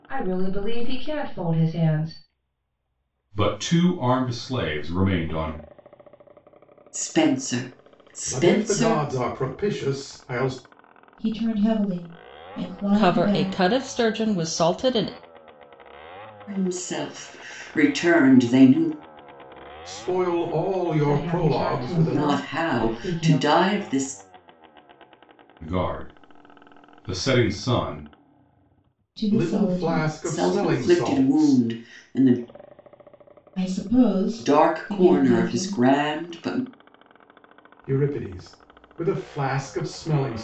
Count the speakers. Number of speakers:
6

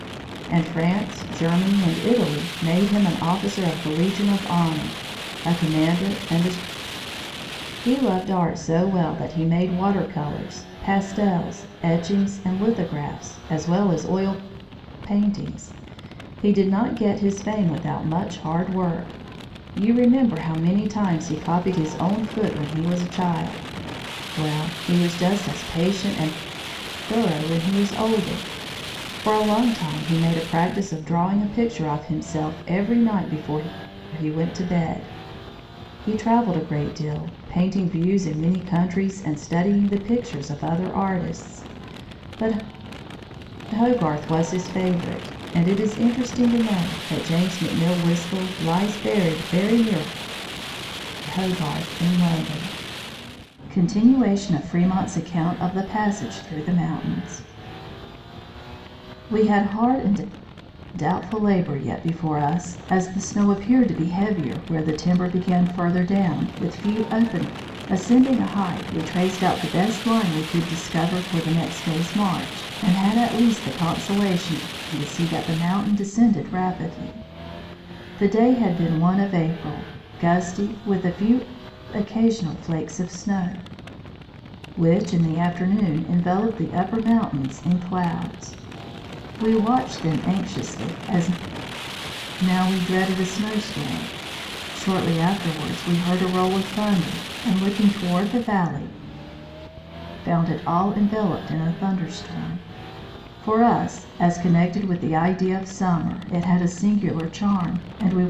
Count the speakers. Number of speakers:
1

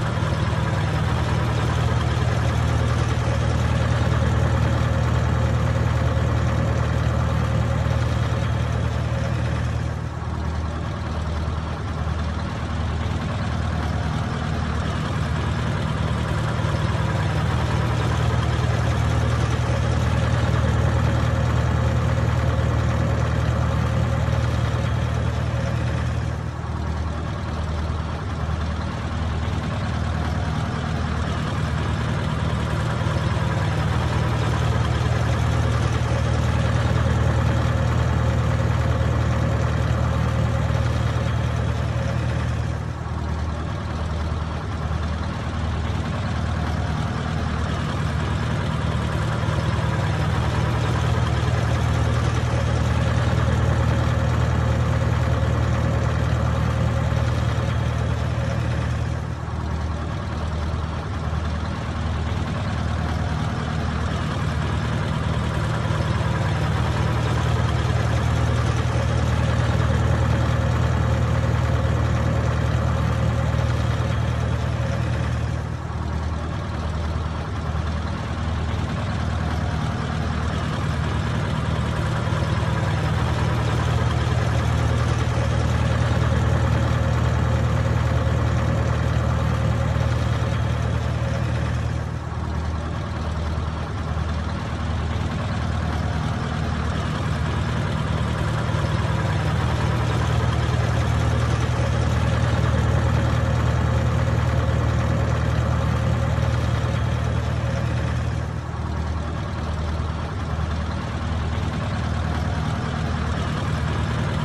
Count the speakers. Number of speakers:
0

